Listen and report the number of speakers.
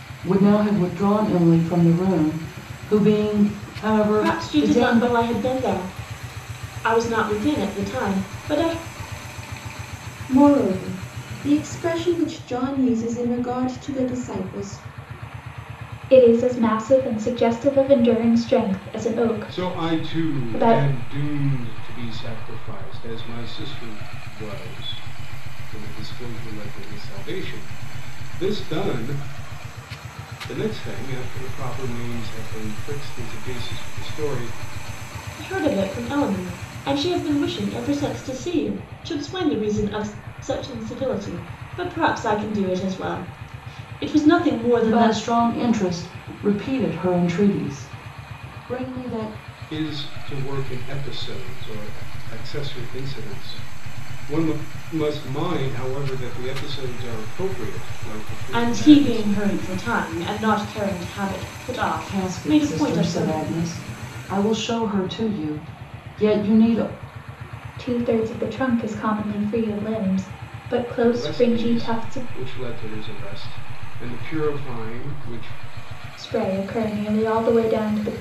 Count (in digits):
5